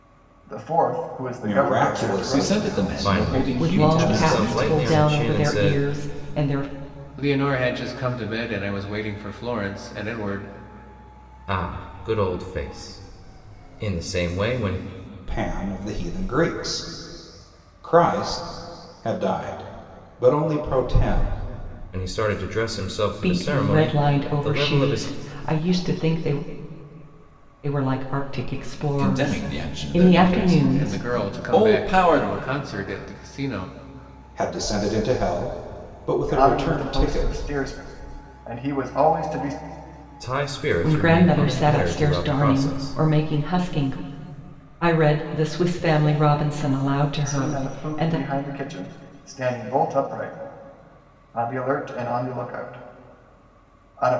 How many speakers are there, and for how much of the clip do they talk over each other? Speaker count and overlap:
6, about 26%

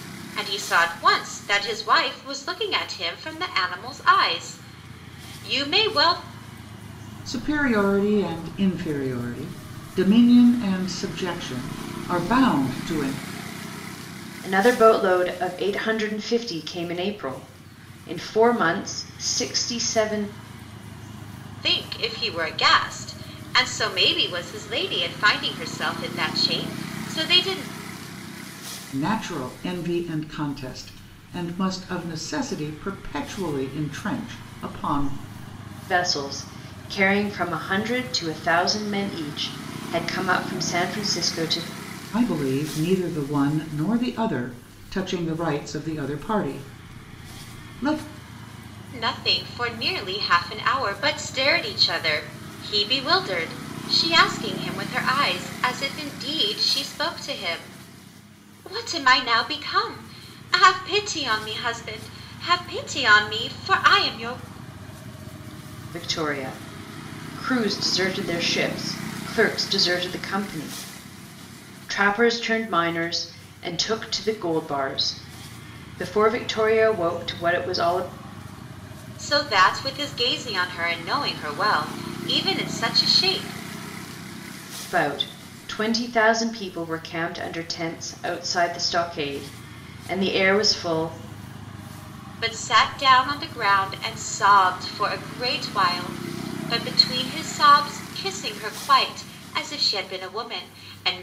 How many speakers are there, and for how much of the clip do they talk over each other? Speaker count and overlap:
3, no overlap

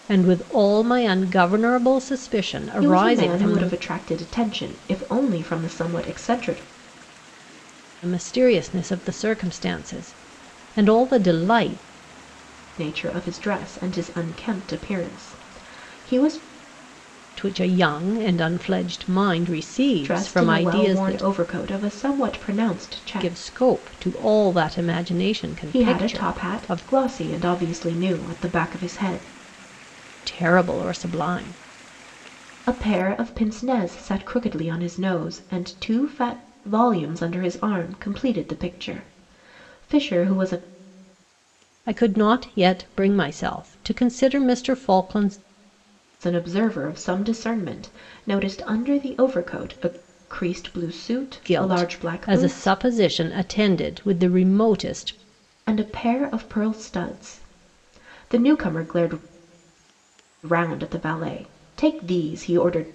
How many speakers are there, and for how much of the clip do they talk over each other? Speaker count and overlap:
2, about 8%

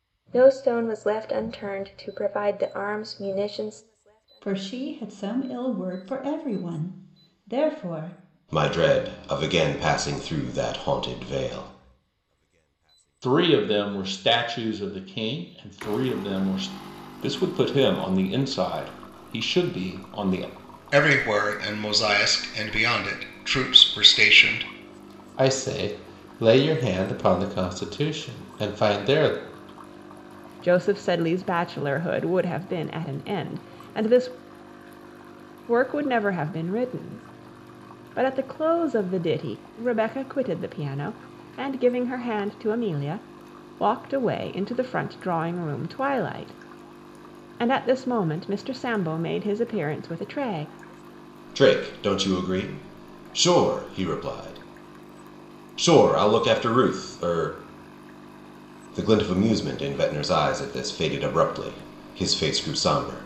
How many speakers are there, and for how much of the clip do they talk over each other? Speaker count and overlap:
8, no overlap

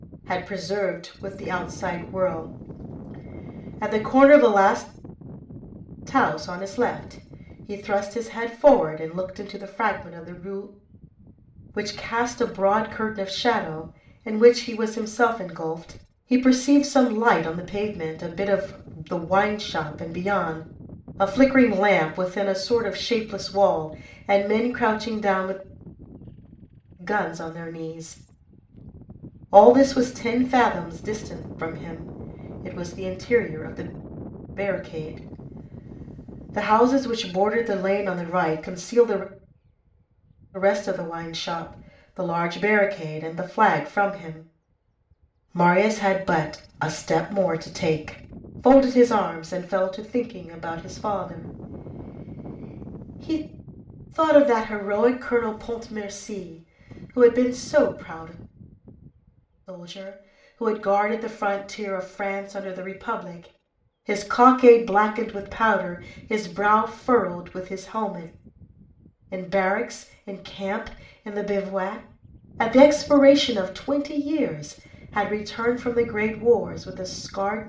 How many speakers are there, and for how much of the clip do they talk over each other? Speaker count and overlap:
1, no overlap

